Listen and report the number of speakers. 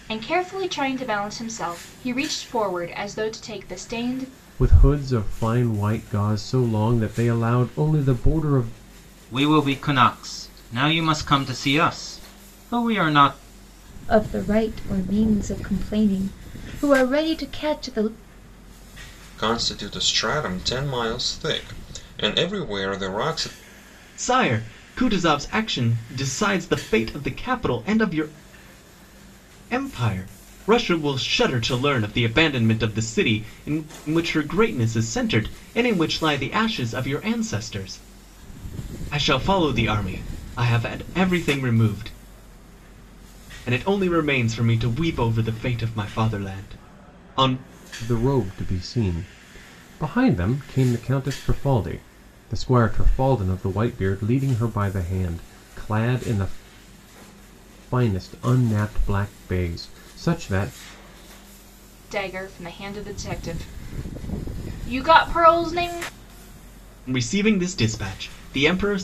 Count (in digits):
6